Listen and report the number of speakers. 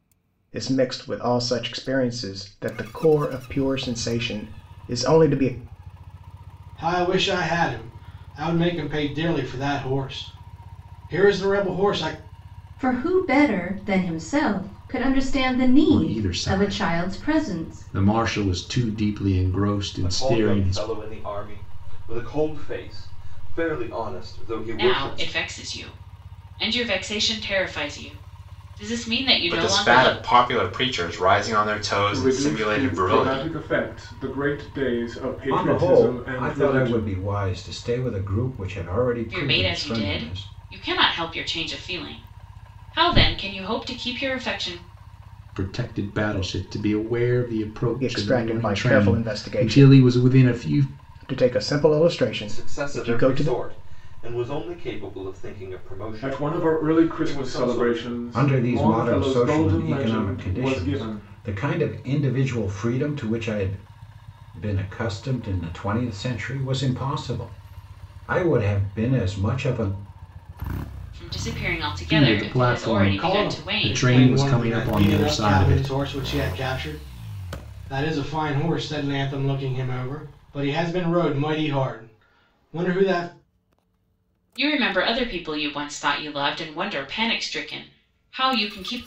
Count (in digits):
9